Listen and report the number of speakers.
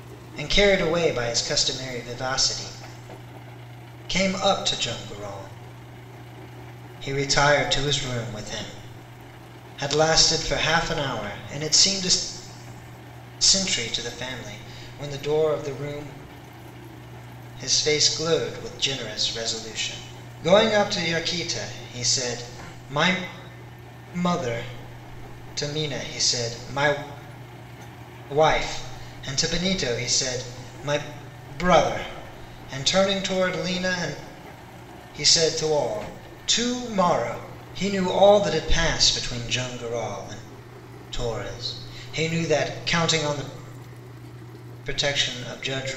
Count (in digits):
1